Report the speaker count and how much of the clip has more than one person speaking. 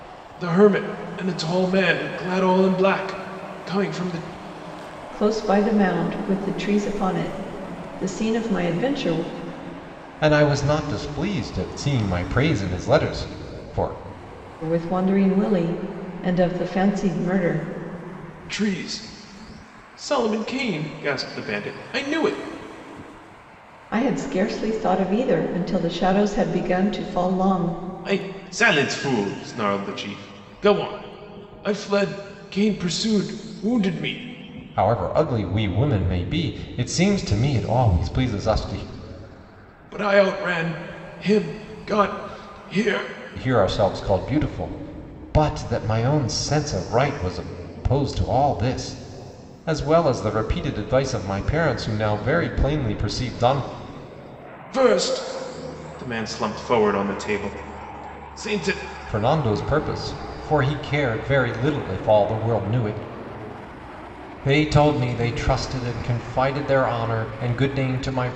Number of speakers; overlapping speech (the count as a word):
three, no overlap